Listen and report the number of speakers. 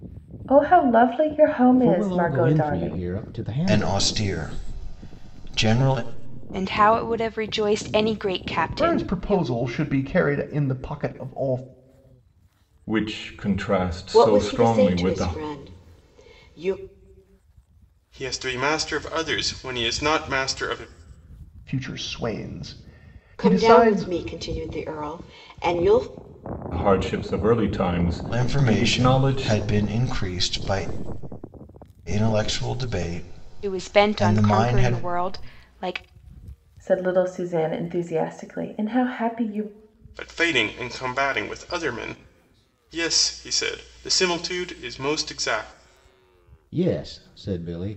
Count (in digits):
8